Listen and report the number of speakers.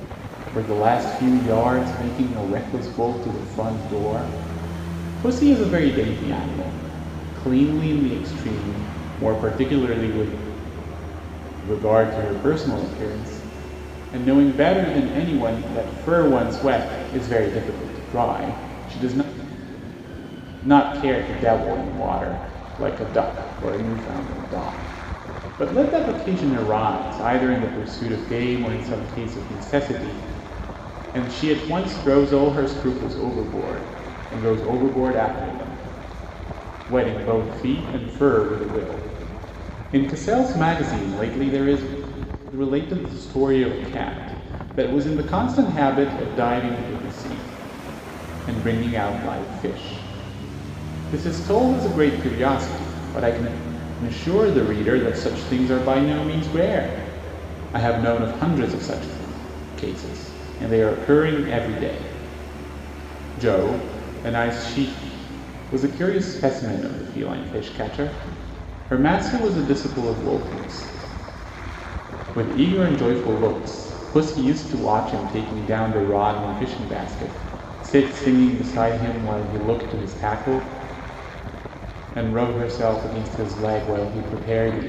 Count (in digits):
1